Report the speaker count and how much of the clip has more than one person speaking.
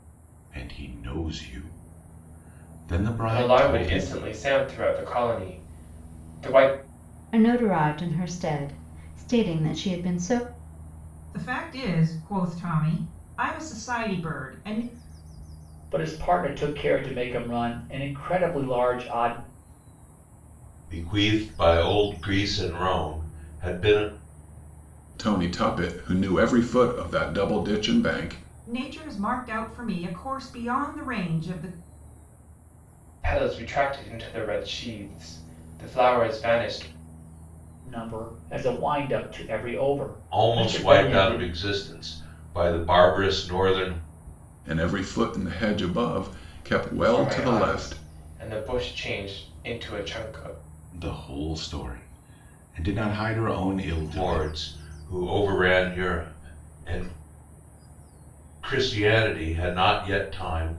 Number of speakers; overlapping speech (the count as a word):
seven, about 6%